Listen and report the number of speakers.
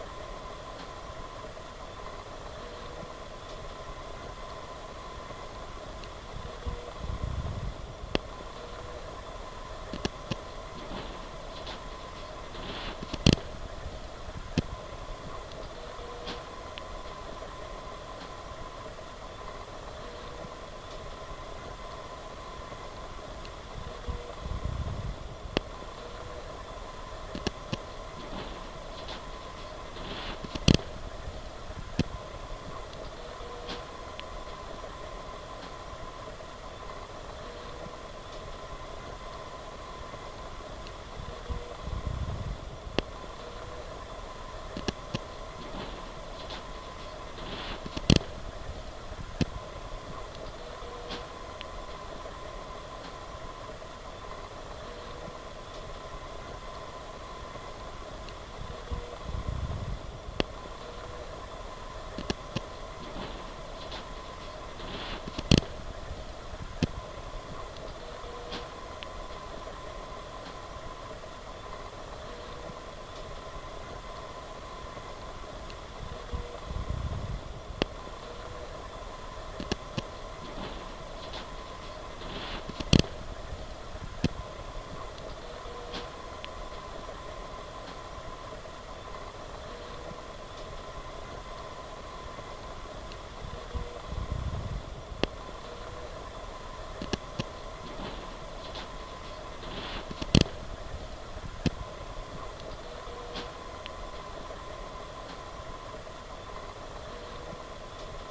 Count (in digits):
0